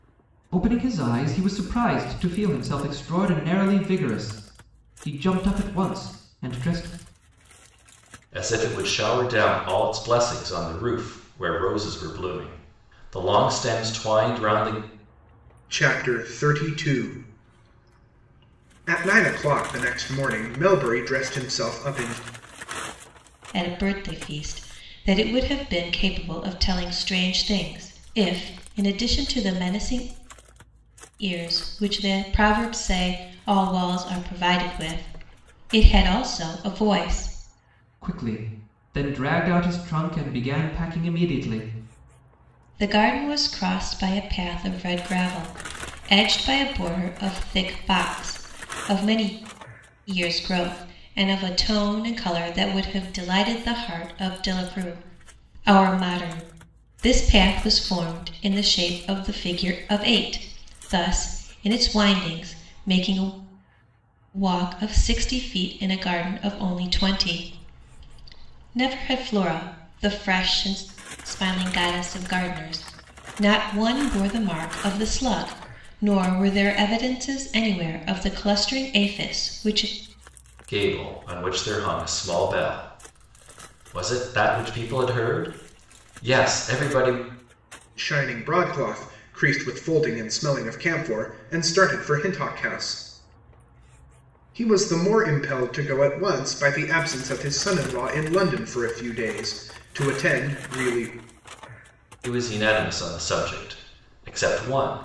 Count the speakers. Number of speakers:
4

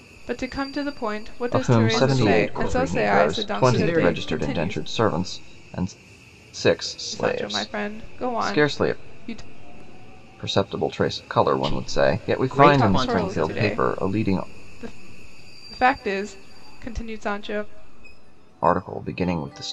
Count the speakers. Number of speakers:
3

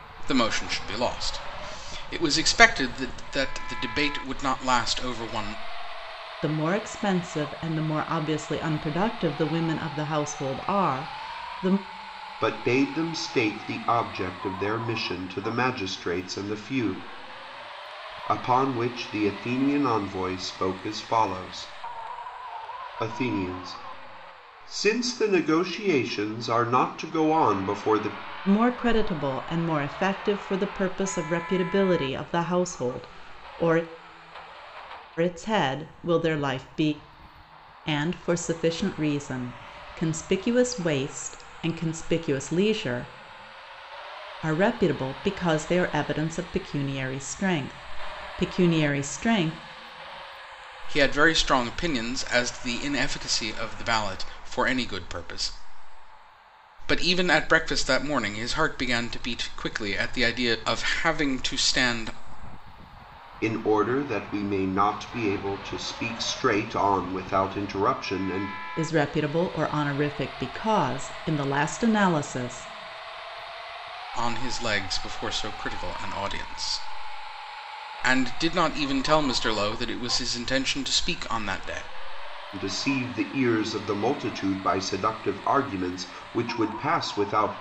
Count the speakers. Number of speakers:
3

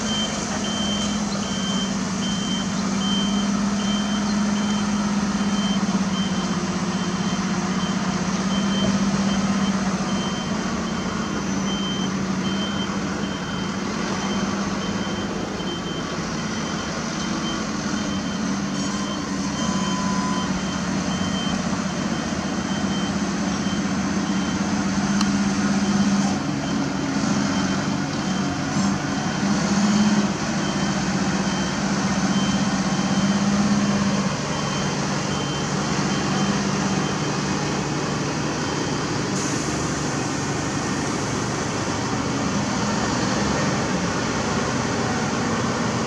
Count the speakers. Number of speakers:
0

